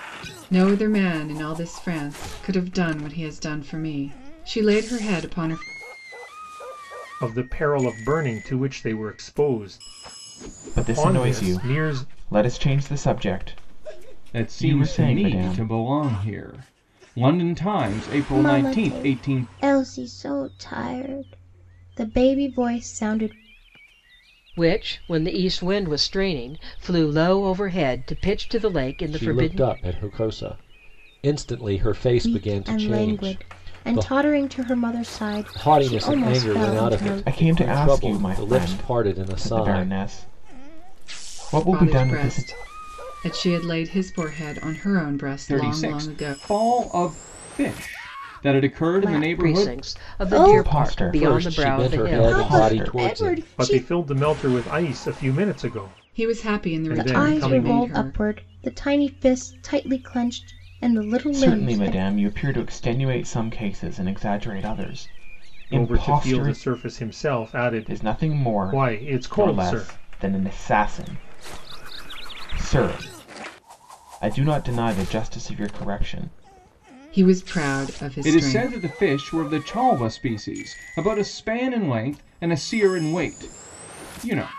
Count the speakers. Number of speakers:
7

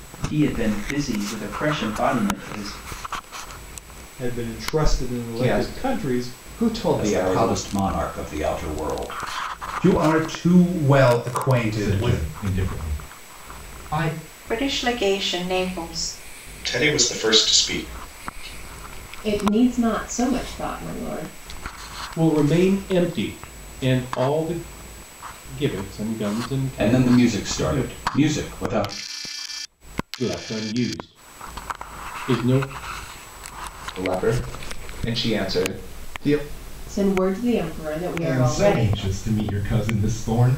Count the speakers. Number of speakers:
10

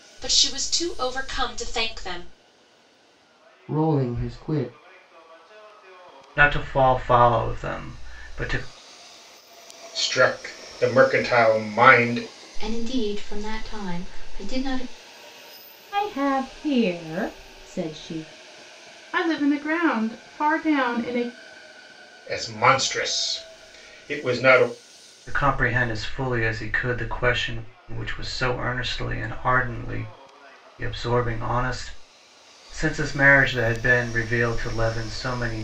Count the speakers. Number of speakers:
7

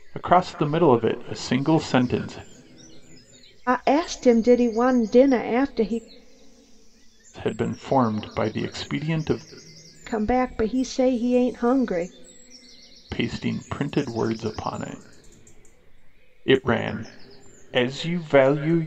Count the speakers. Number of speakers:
2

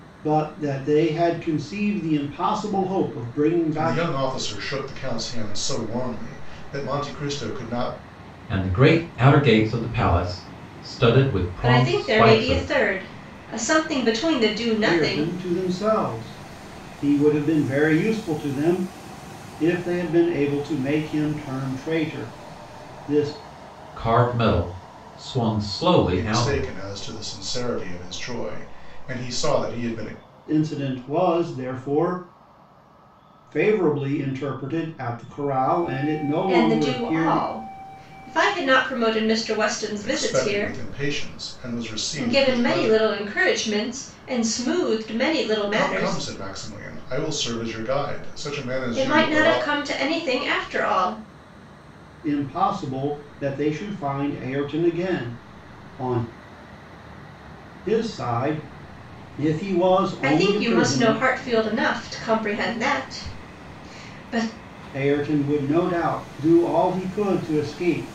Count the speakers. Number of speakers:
4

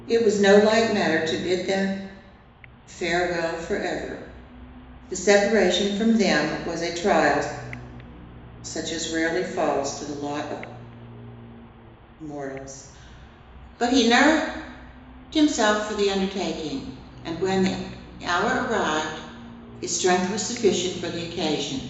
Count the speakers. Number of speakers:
1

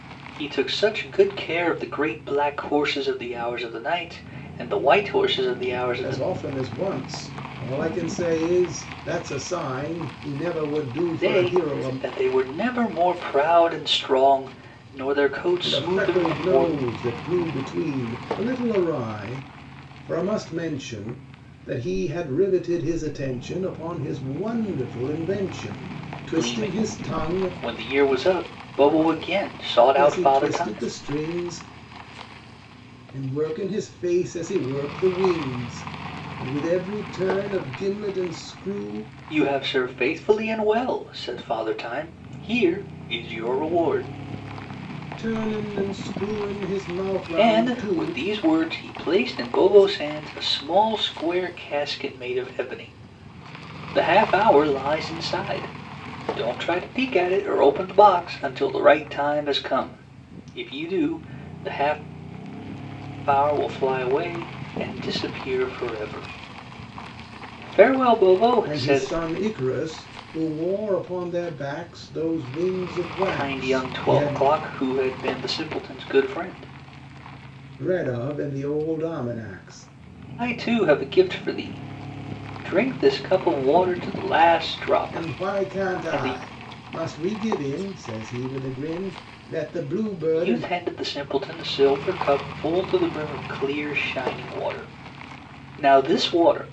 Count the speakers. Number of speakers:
2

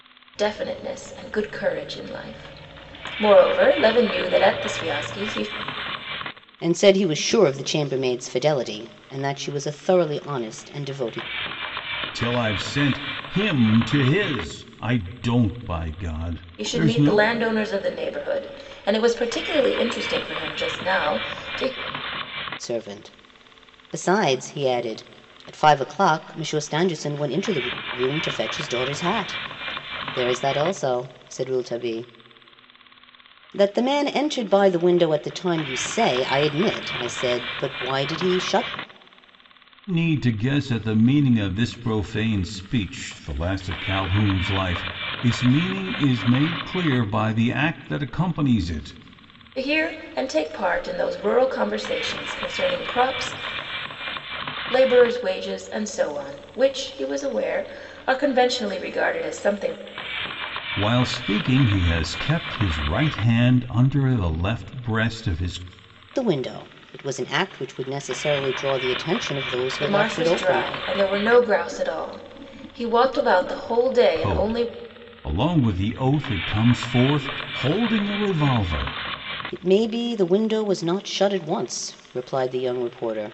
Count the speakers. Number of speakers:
3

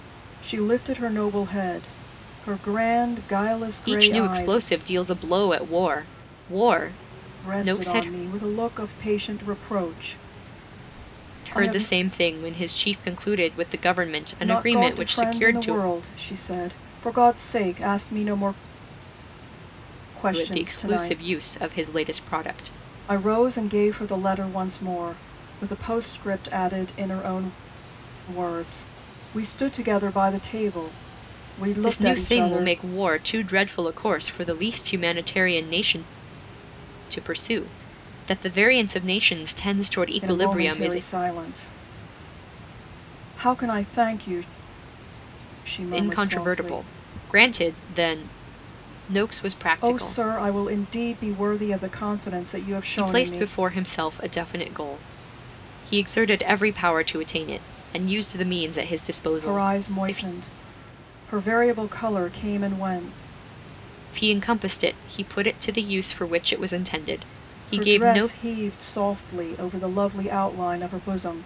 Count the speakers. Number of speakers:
2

